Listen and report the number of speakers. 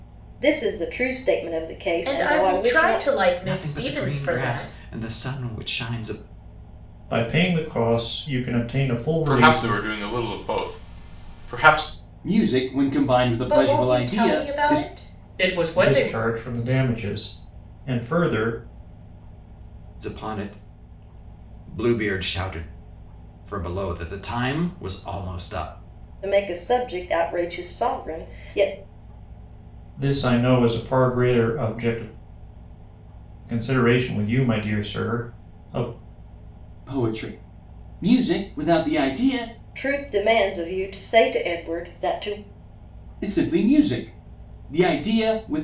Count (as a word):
six